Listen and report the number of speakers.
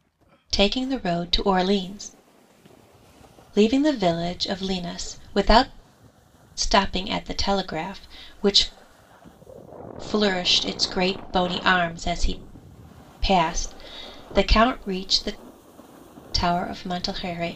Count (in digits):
1